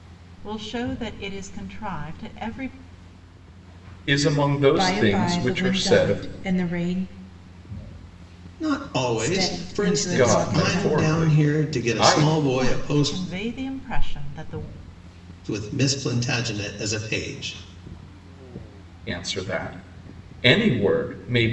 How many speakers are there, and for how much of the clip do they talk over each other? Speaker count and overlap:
4, about 25%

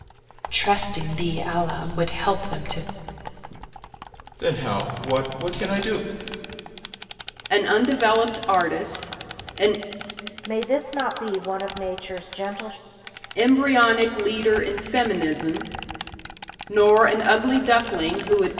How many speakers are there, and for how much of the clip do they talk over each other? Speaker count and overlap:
4, no overlap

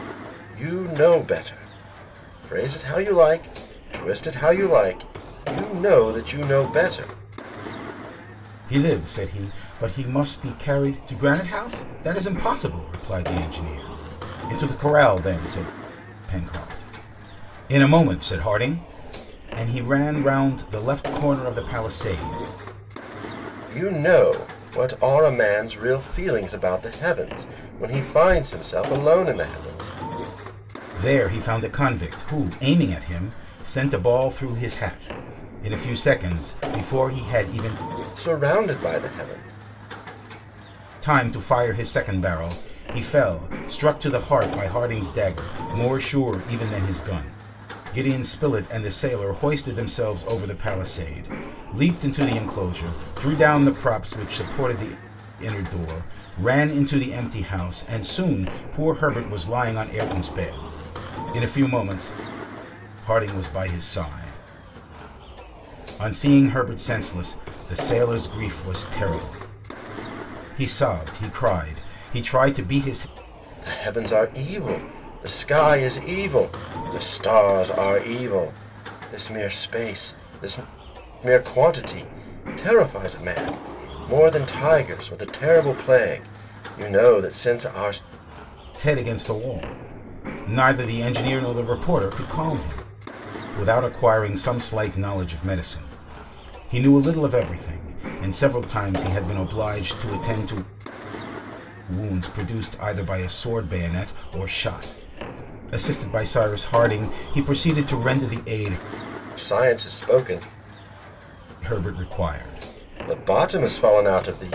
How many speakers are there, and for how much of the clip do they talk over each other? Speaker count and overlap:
2, no overlap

